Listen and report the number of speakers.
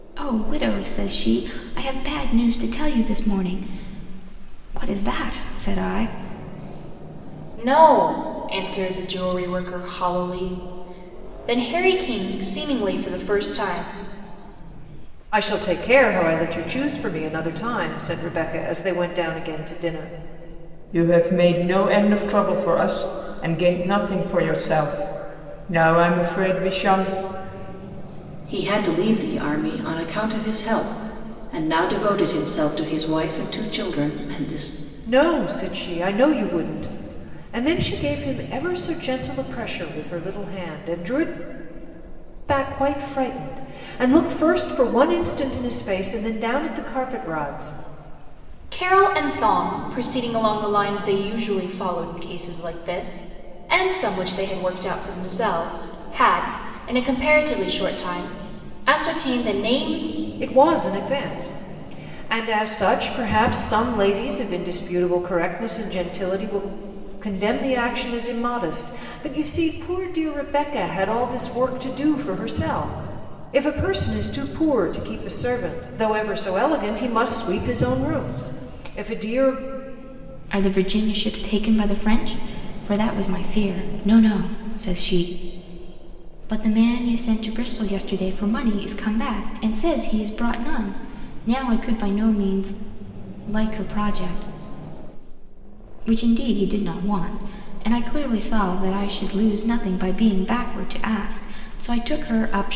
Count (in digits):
5